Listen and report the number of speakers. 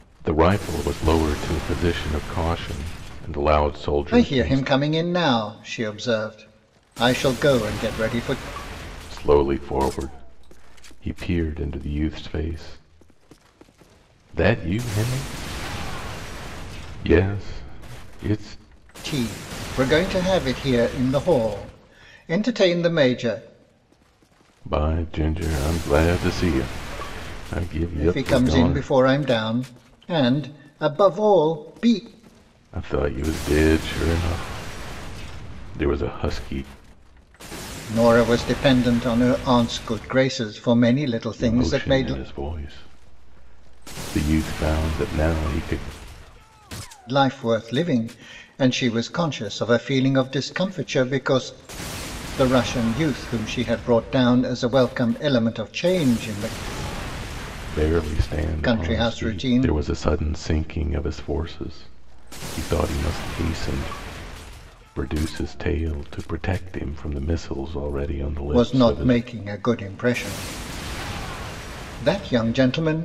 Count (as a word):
two